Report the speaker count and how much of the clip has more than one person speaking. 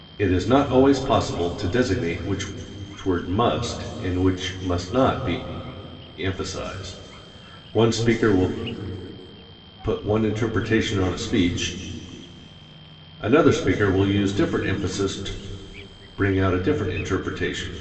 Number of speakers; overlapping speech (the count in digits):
1, no overlap